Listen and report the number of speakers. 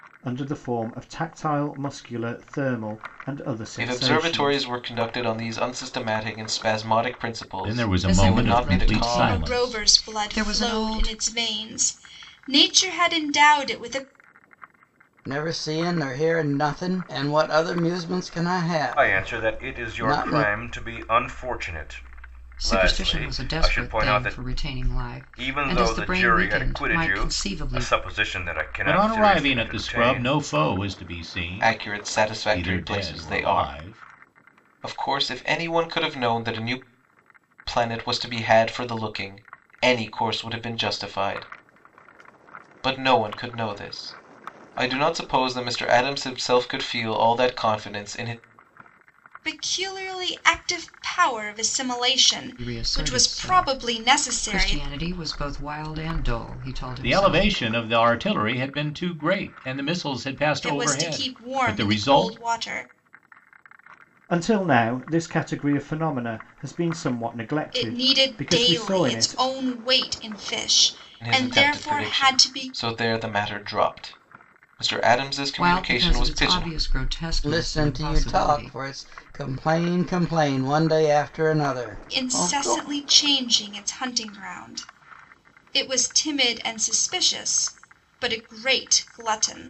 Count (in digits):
7